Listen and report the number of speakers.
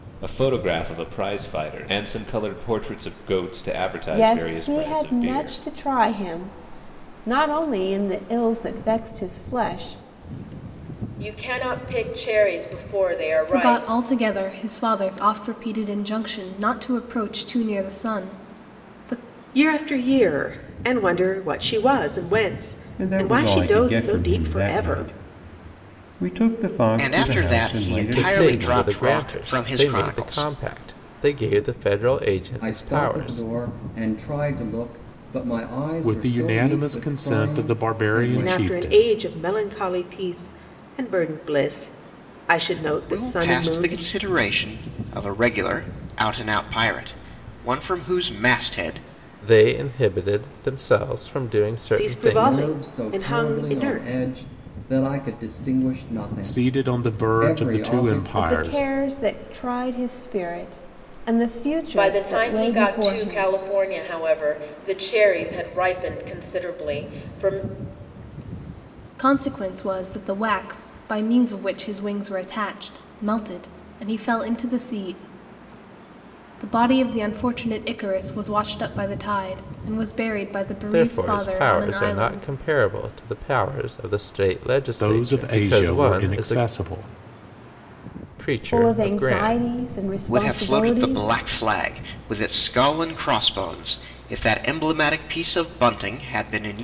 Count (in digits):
10